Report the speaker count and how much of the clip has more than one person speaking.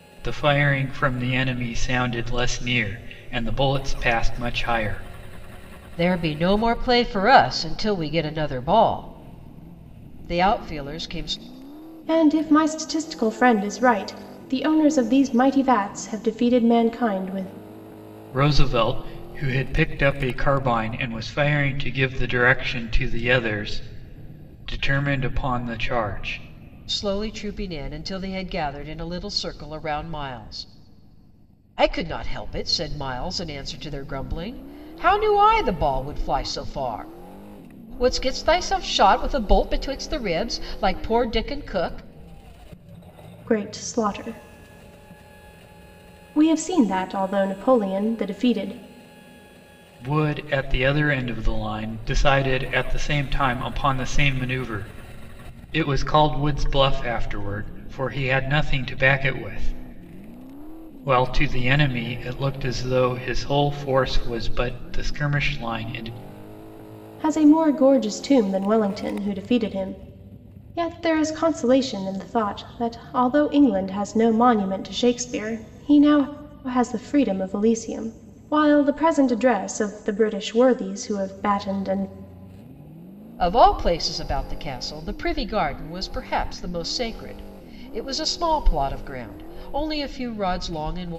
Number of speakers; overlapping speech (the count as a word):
three, no overlap